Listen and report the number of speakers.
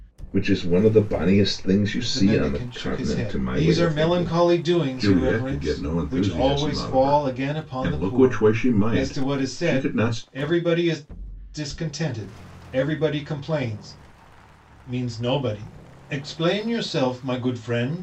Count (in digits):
2